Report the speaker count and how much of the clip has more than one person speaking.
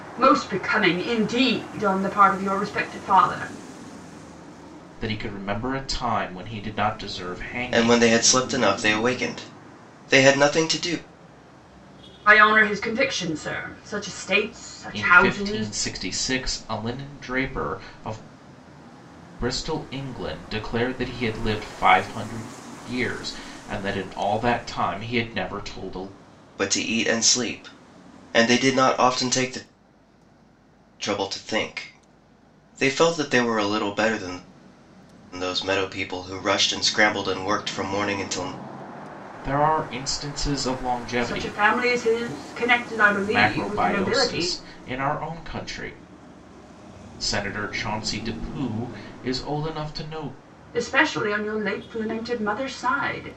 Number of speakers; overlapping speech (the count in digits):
3, about 5%